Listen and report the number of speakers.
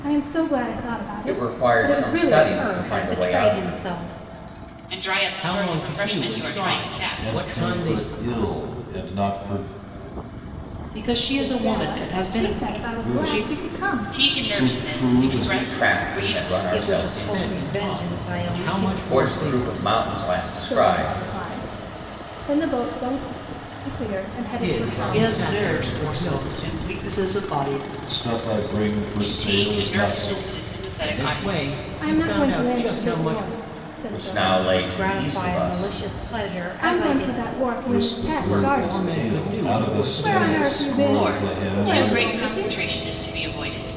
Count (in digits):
7